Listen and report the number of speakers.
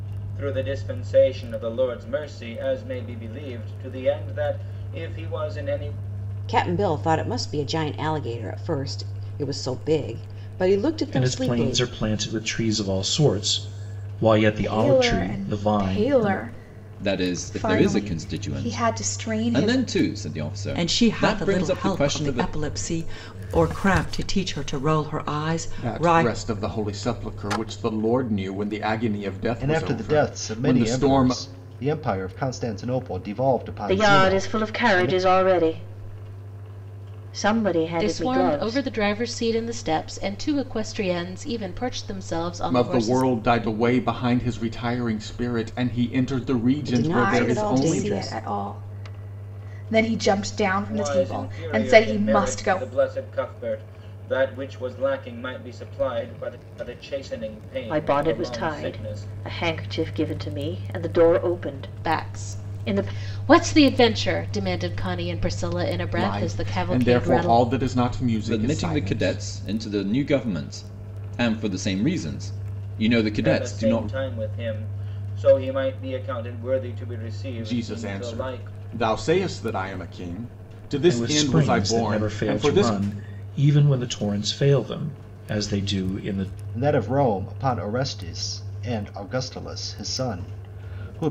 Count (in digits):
10